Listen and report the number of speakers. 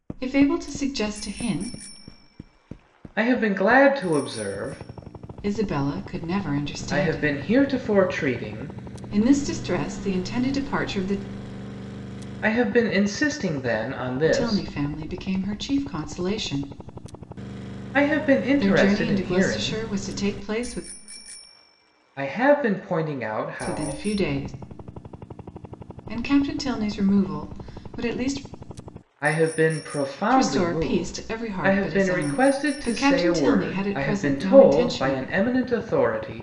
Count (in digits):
2